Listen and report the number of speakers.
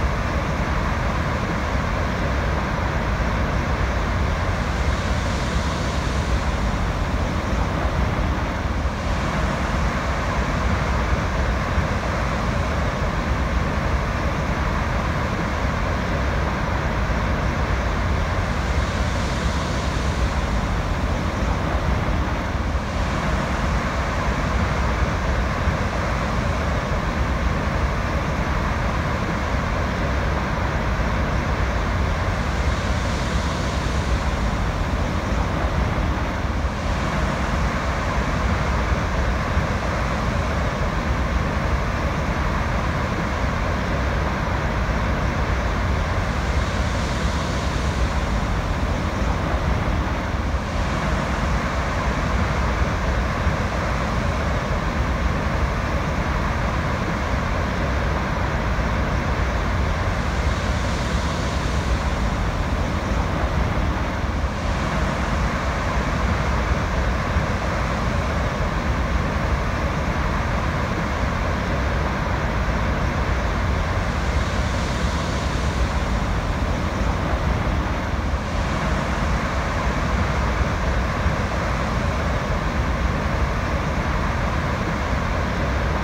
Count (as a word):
zero